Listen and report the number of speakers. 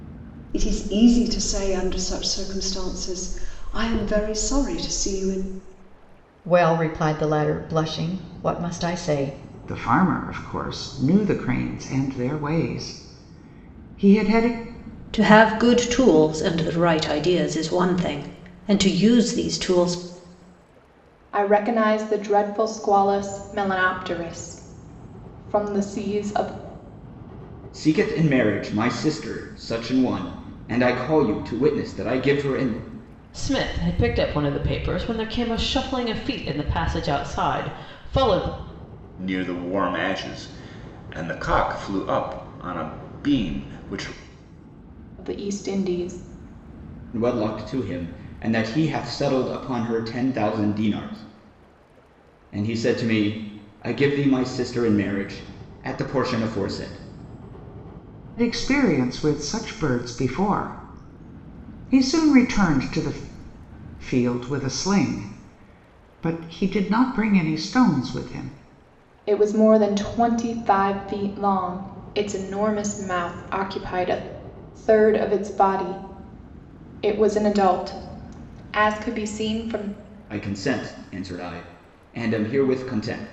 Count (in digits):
8